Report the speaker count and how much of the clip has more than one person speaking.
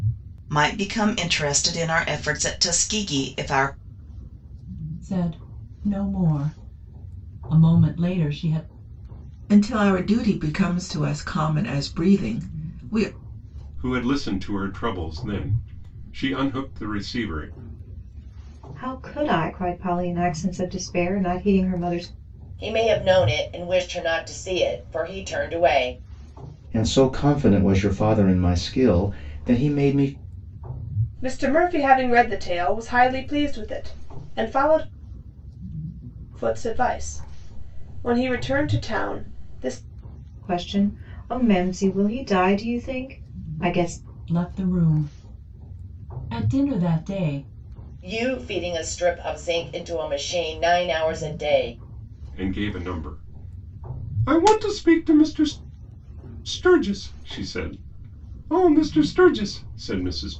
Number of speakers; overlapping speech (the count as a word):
eight, no overlap